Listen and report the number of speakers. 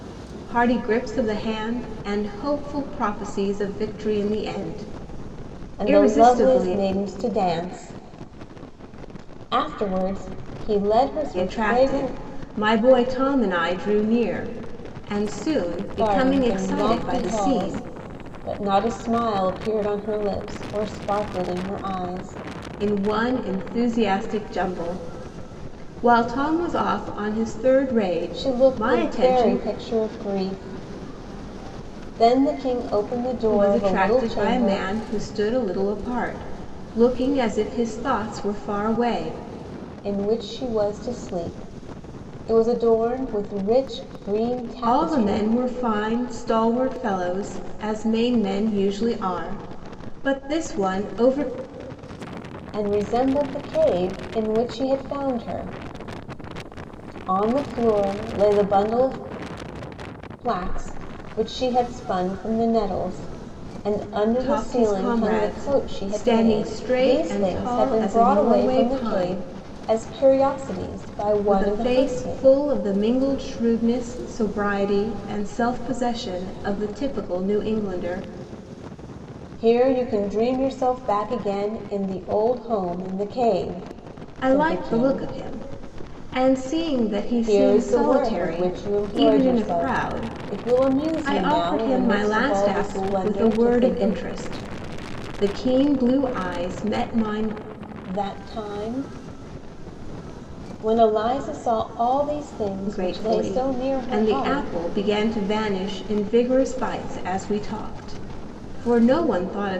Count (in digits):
2